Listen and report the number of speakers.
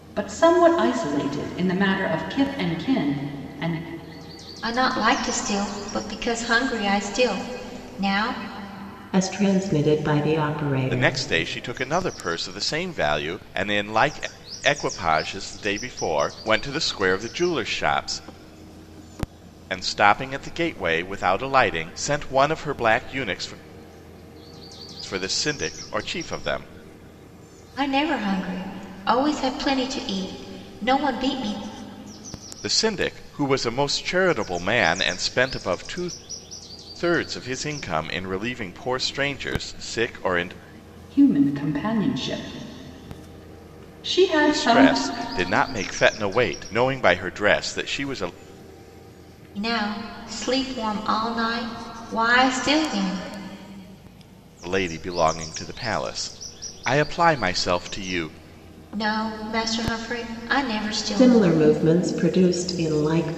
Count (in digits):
4